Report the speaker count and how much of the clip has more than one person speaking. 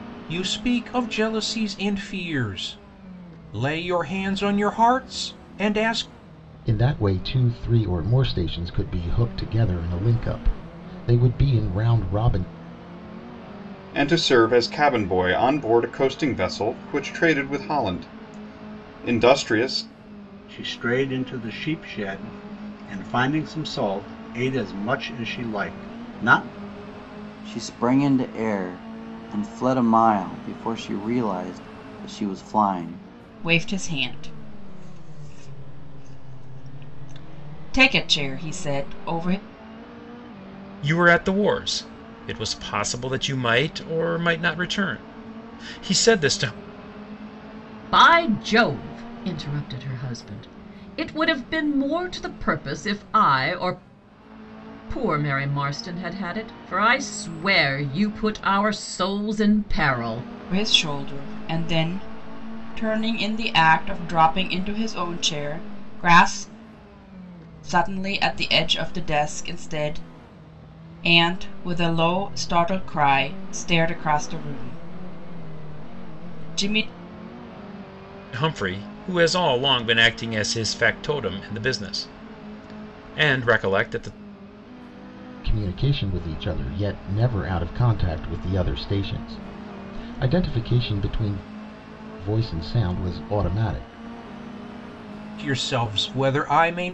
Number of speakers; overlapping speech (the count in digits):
8, no overlap